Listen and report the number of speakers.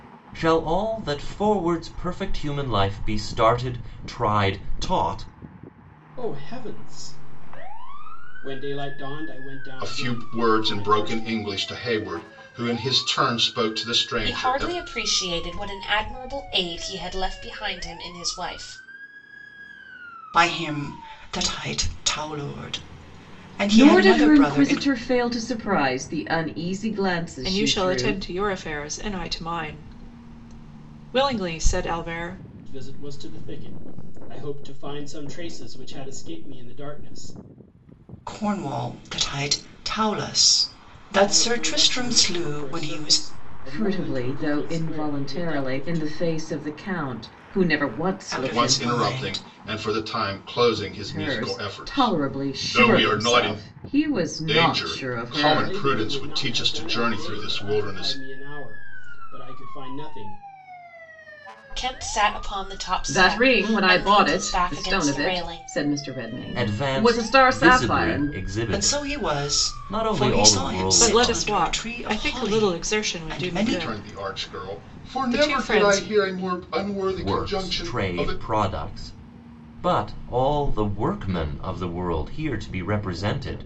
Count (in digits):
7